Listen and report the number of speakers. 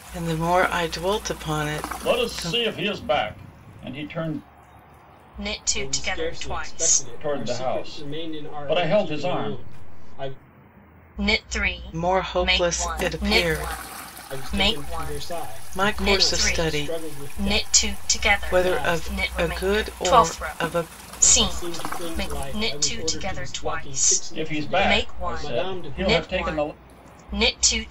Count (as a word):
four